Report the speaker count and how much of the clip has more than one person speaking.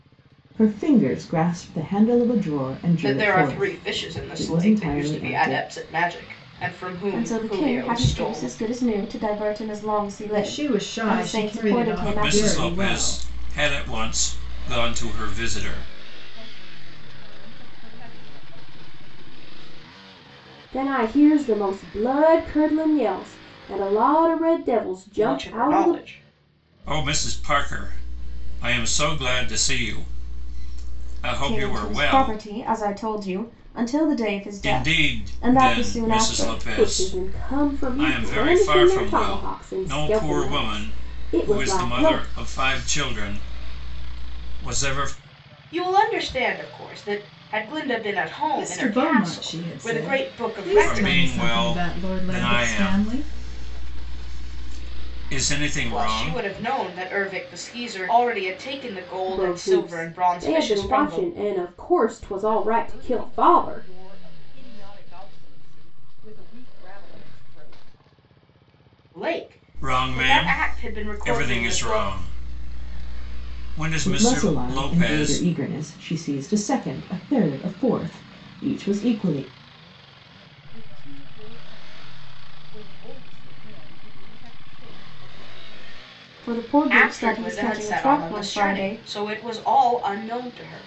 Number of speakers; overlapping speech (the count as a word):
seven, about 35%